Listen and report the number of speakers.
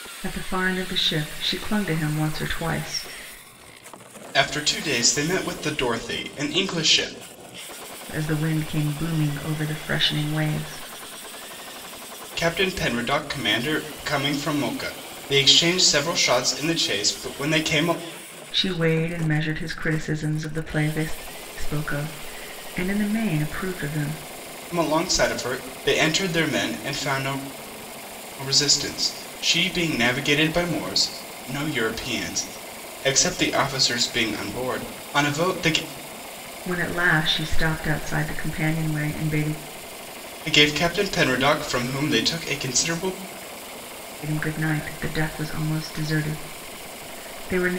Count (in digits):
2